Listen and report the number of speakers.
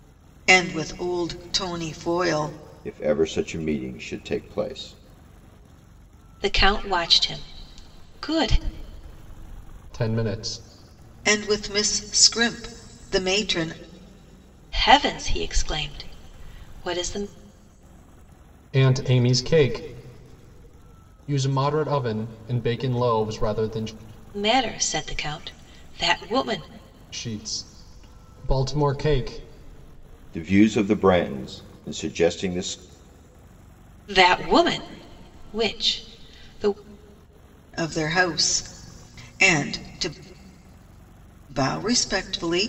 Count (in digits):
4